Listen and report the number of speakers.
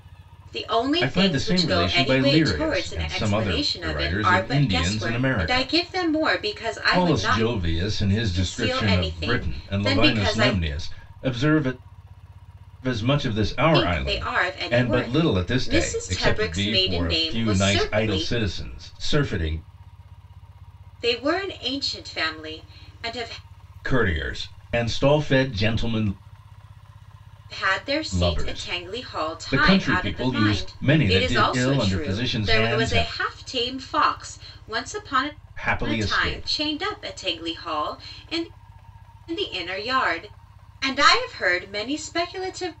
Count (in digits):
2